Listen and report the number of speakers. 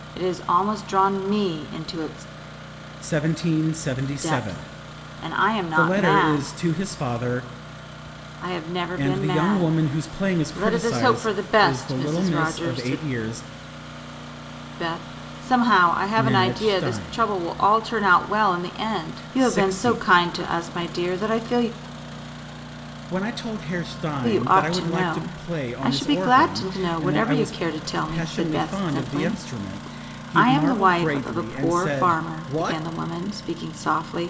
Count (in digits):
2